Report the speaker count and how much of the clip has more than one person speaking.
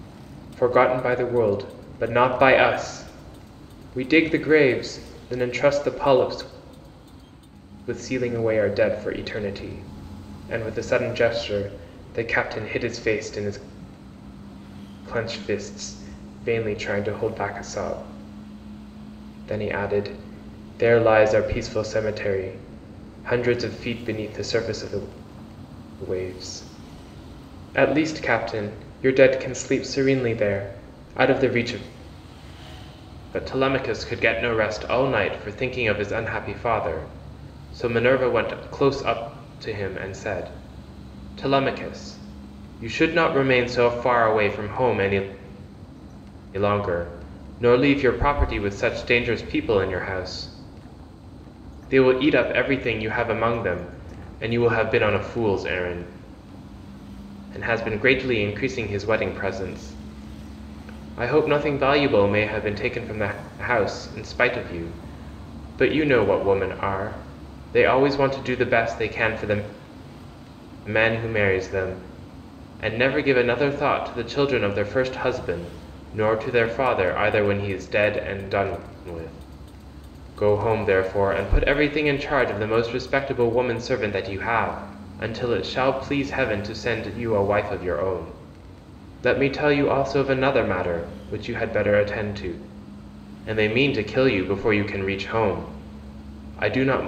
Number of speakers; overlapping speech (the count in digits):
1, no overlap